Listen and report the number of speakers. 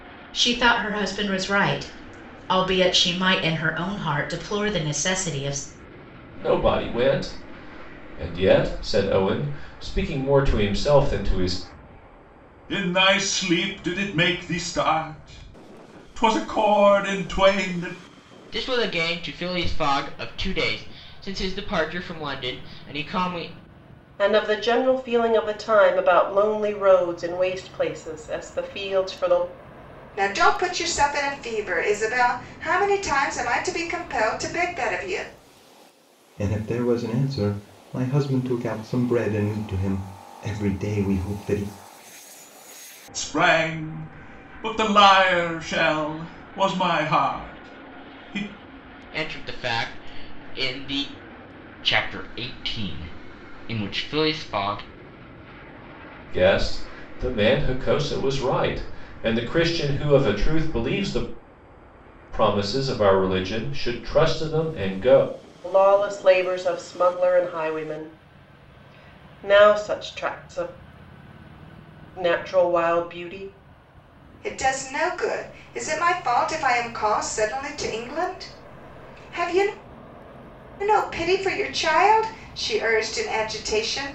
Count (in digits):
7